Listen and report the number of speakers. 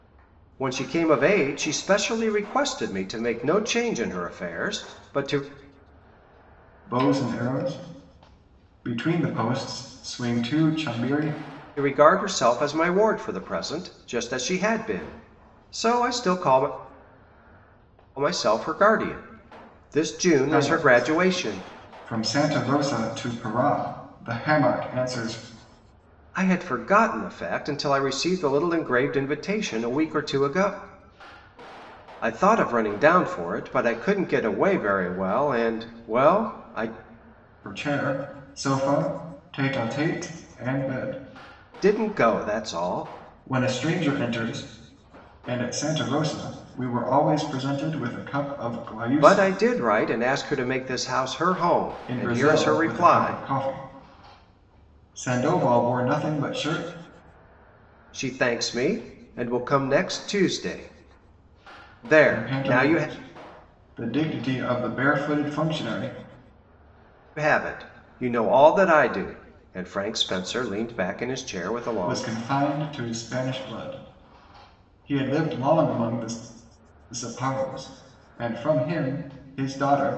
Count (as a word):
two